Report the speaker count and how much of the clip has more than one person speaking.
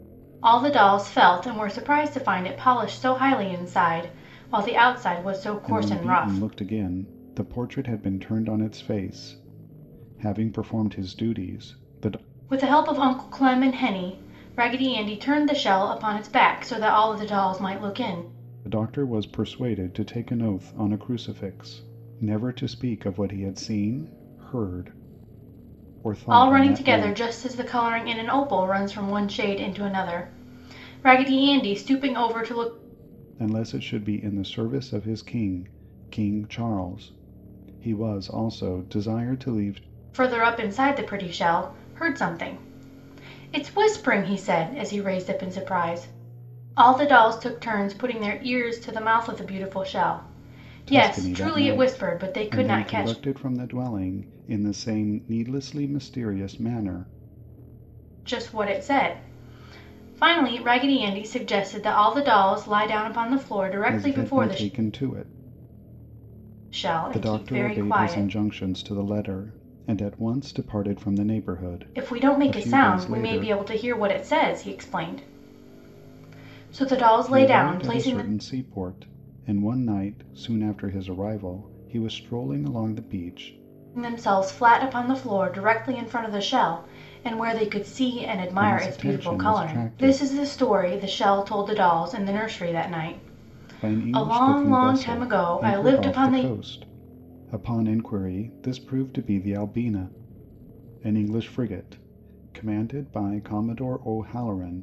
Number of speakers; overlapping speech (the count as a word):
two, about 13%